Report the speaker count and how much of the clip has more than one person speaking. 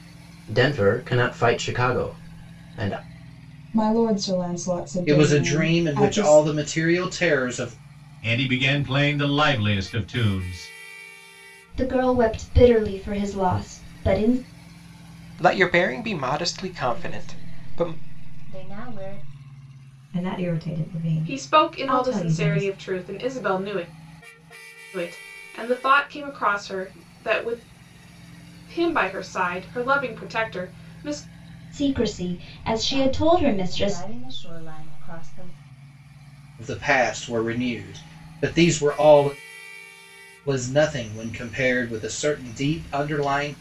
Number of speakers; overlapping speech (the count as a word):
nine, about 12%